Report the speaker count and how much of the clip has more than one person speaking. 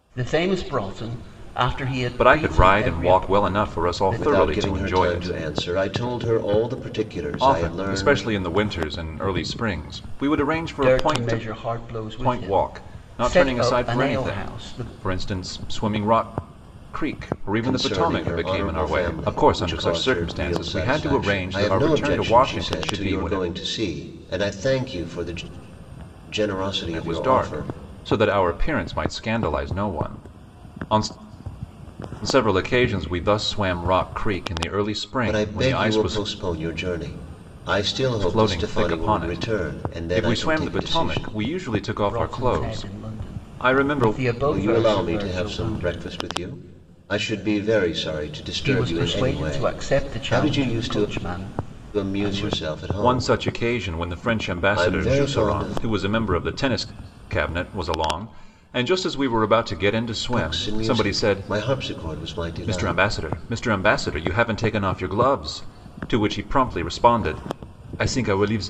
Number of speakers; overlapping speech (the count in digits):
3, about 43%